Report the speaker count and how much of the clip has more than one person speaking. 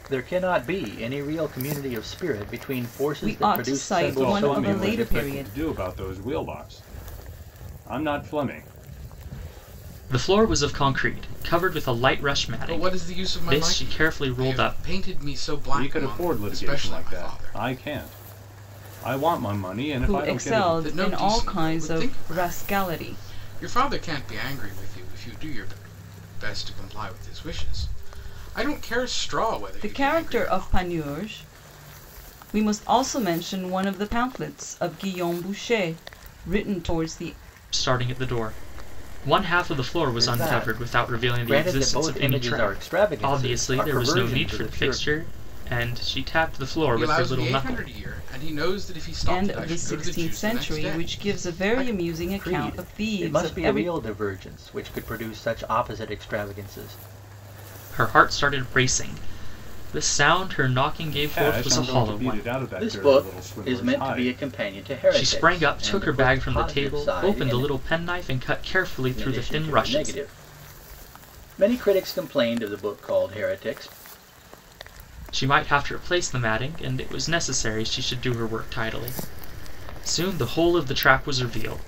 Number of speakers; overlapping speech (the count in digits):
5, about 34%